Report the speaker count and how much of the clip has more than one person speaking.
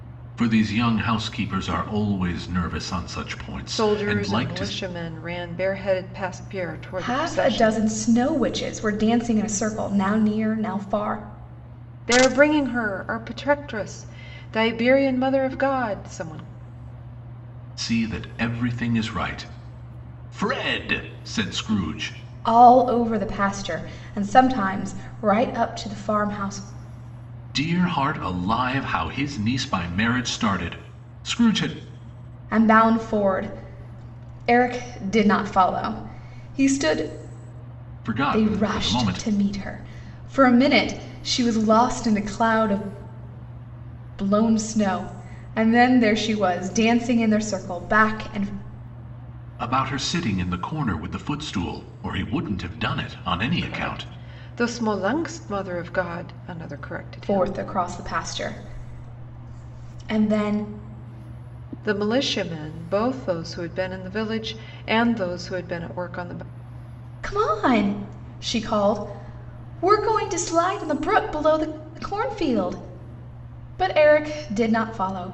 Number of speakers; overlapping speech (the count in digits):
3, about 5%